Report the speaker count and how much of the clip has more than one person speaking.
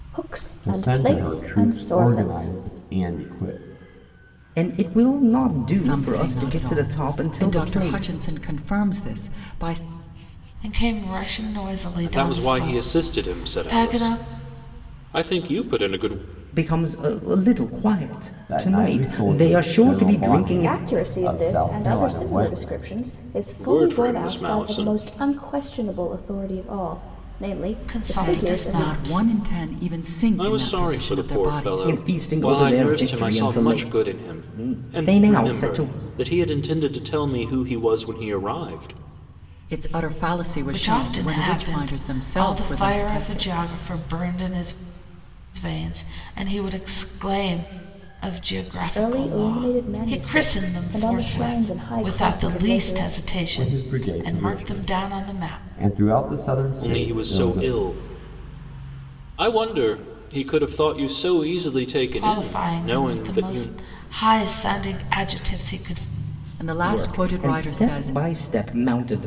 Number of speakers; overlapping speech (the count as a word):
six, about 46%